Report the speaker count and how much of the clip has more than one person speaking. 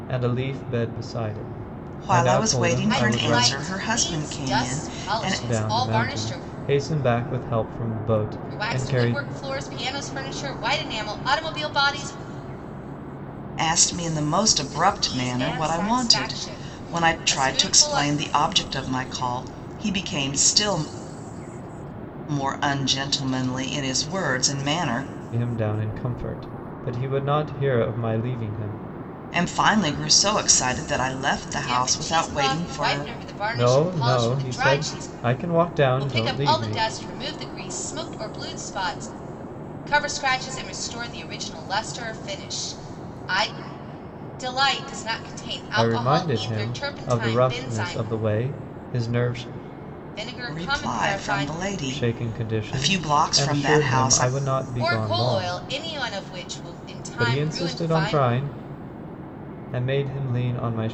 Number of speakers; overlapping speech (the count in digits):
3, about 34%